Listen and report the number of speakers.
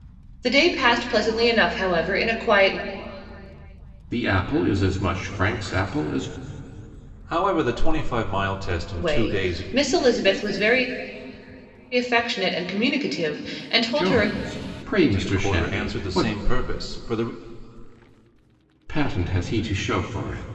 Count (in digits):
3